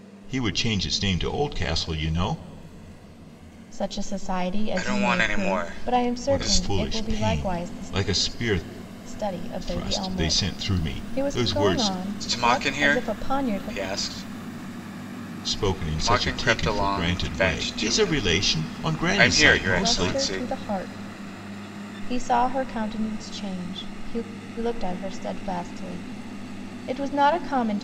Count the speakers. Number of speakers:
3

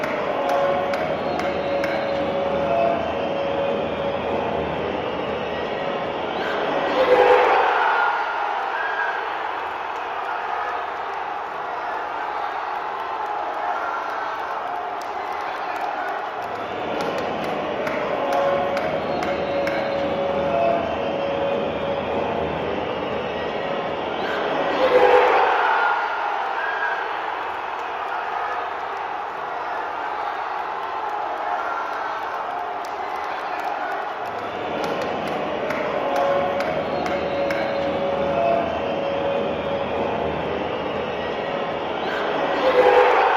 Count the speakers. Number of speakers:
0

